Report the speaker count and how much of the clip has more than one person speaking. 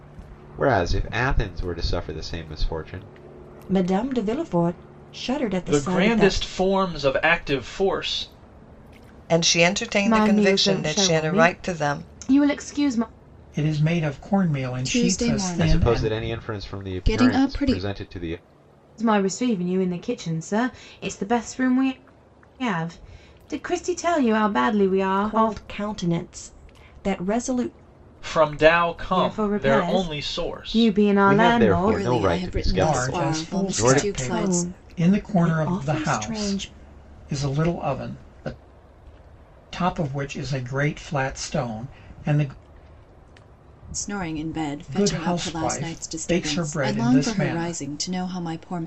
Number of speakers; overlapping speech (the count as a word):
seven, about 34%